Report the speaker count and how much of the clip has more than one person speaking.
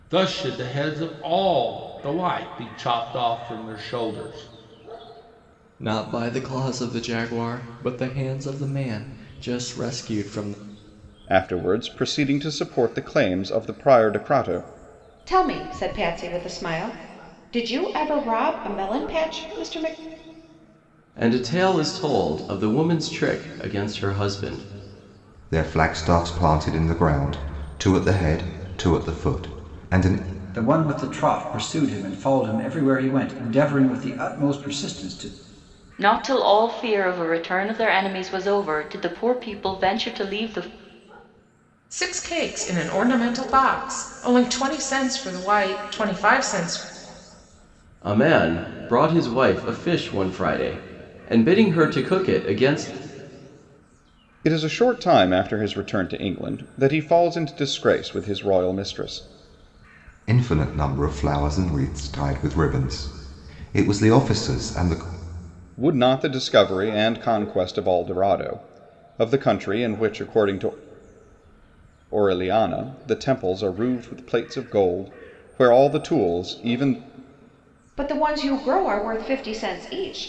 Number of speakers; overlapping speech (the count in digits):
9, no overlap